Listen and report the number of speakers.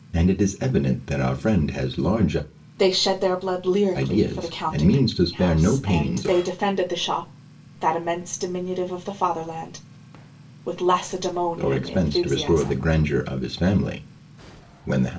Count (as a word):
two